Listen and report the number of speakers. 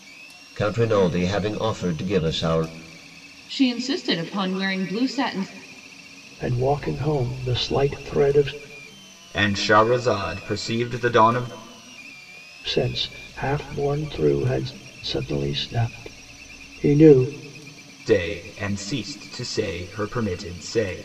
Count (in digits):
4